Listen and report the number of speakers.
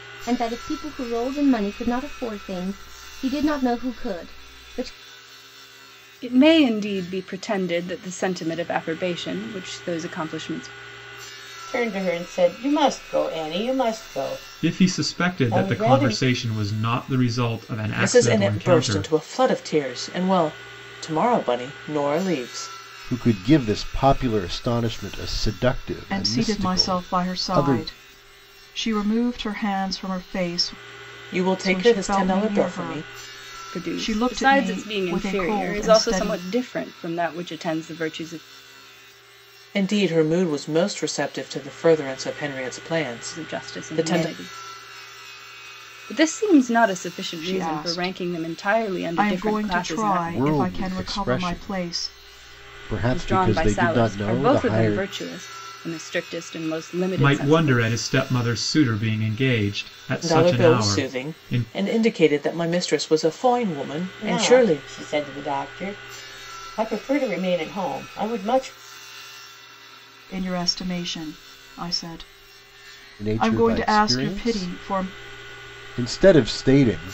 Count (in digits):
7